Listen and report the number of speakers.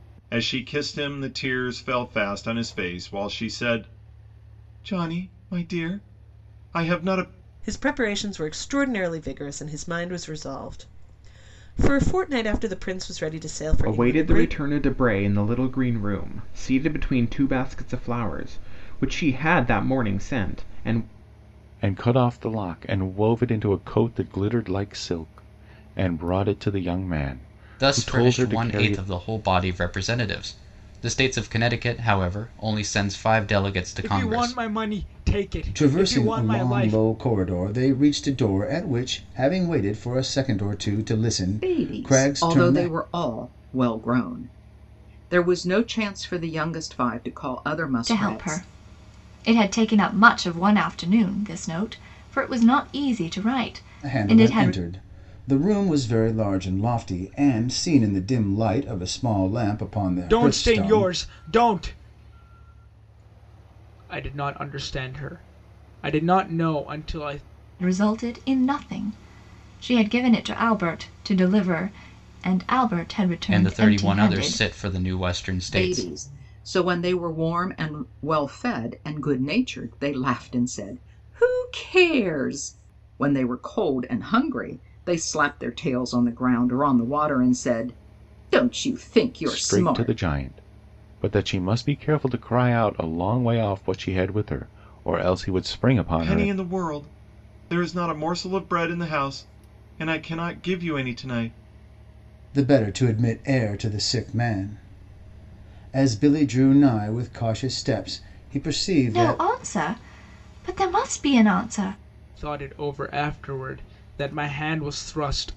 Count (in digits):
9